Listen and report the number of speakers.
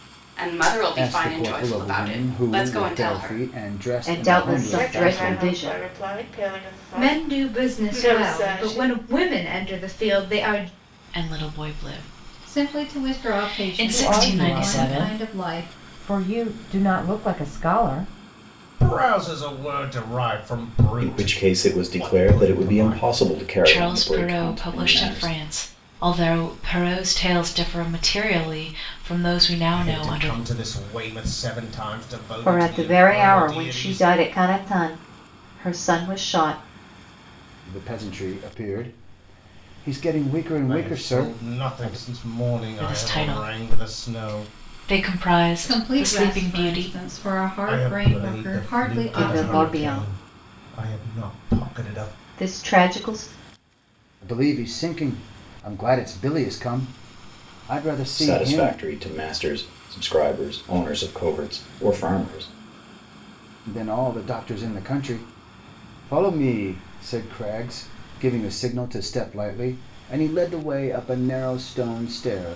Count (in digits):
10